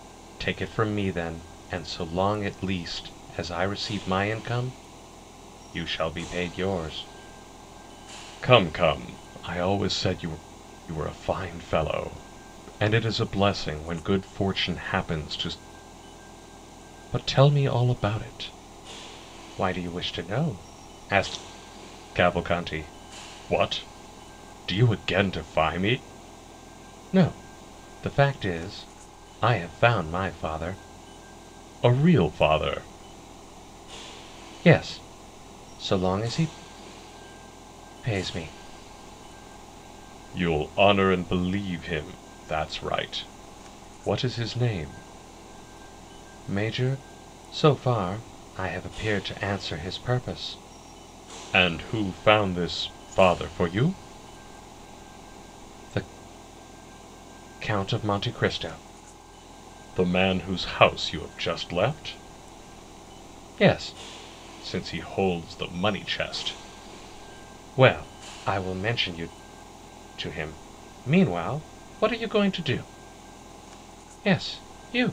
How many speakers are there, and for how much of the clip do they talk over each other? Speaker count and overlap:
one, no overlap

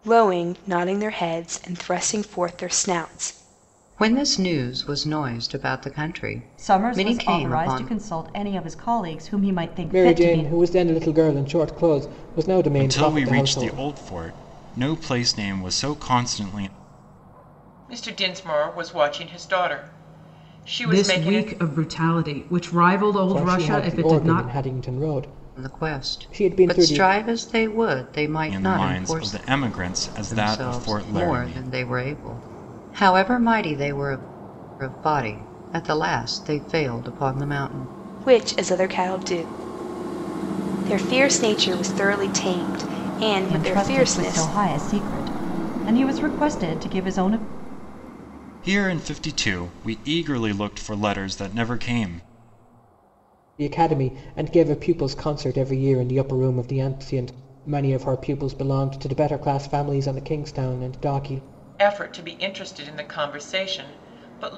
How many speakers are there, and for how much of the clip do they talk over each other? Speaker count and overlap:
seven, about 16%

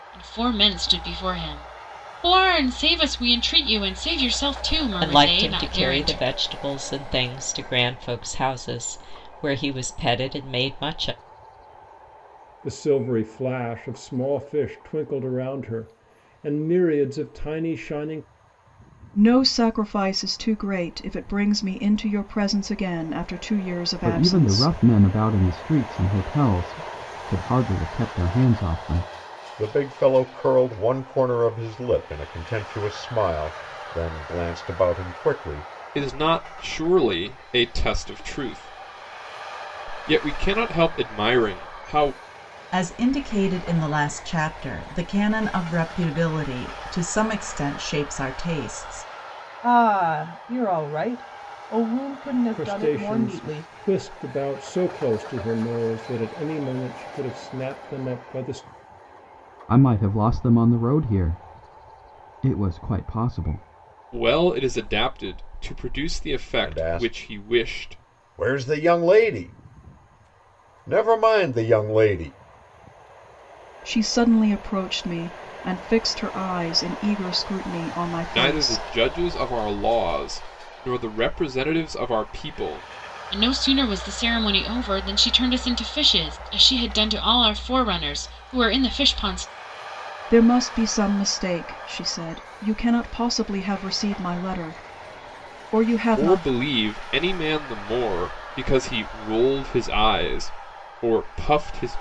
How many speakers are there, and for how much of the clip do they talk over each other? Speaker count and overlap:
nine, about 6%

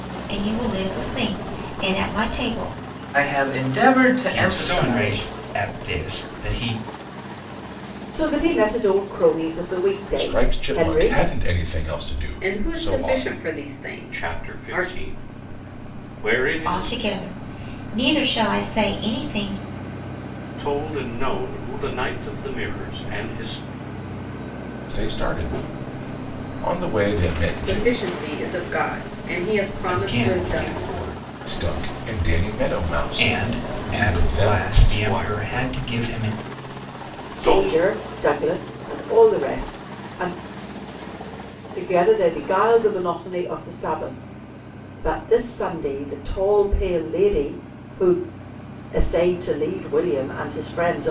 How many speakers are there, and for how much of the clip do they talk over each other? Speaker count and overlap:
seven, about 17%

